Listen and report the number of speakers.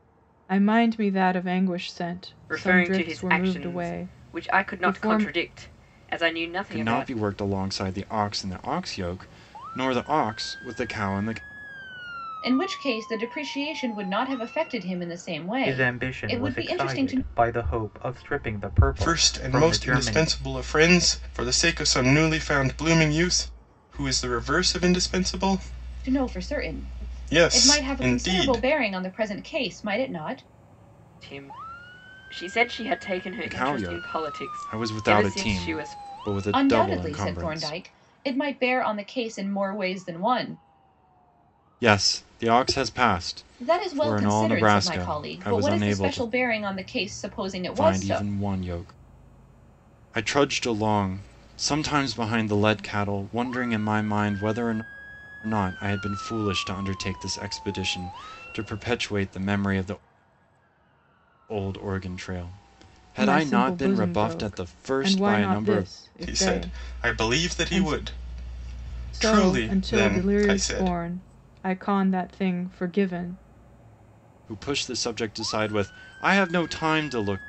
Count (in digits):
6